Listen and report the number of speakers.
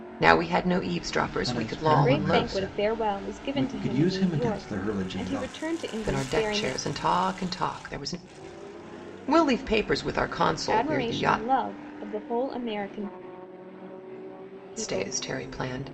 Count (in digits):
3